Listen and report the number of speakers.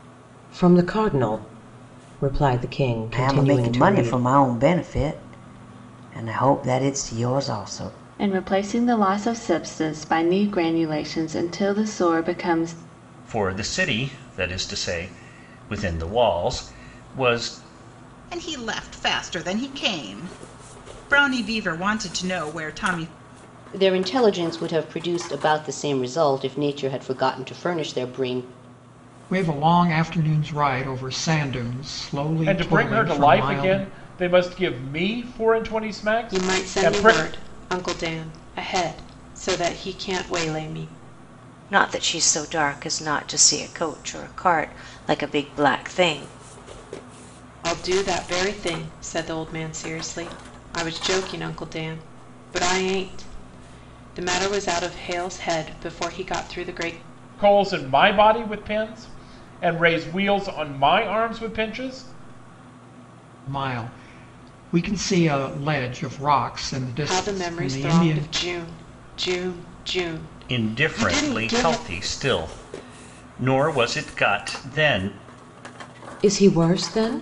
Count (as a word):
ten